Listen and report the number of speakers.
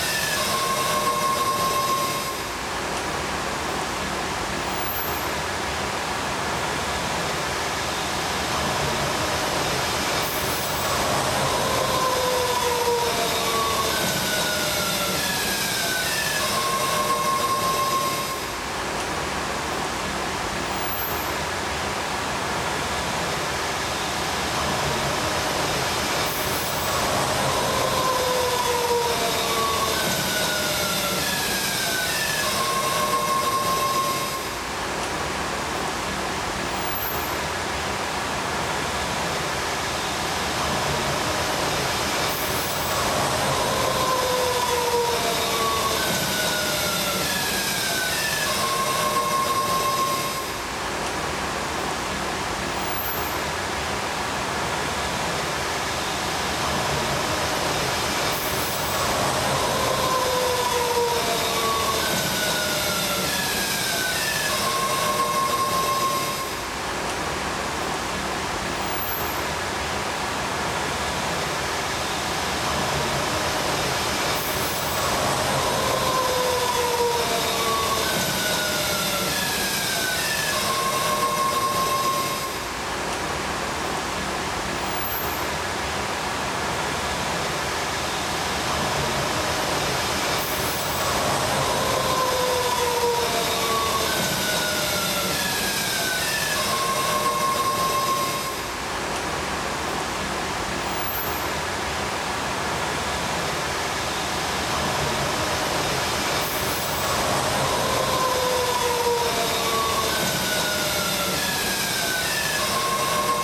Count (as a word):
zero